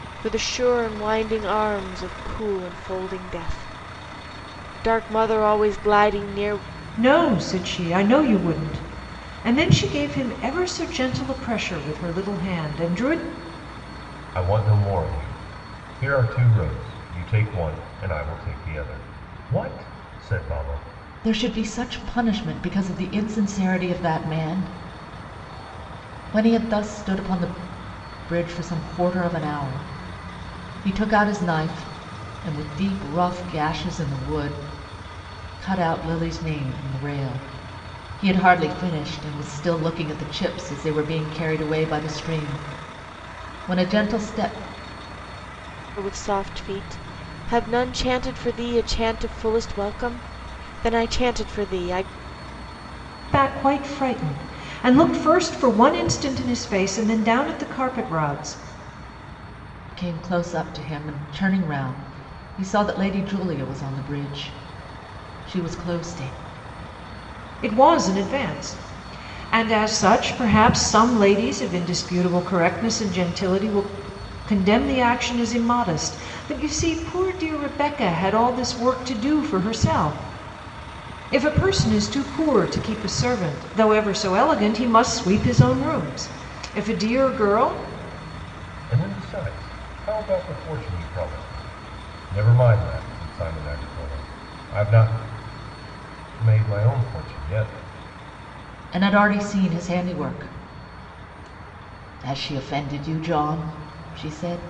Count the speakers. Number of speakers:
four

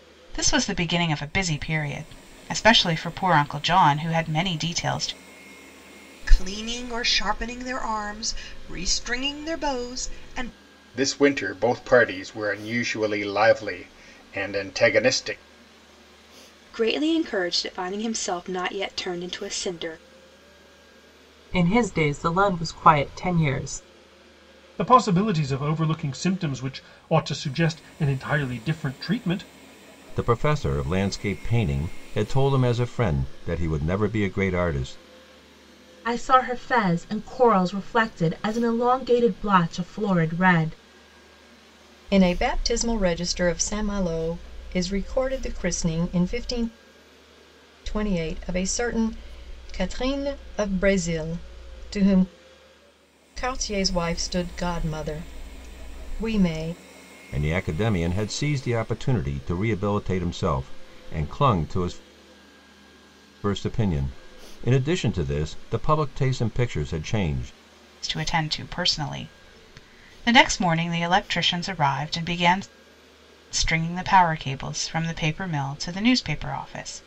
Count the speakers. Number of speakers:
nine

